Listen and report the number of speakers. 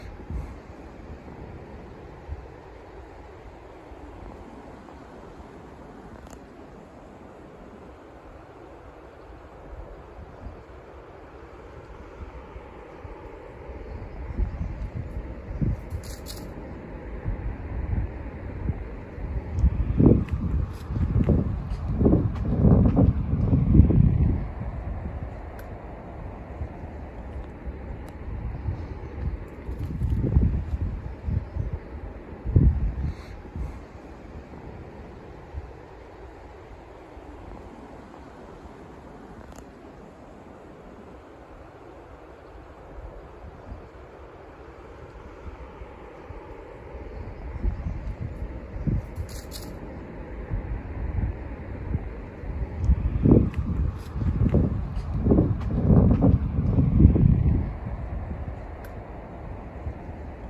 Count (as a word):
zero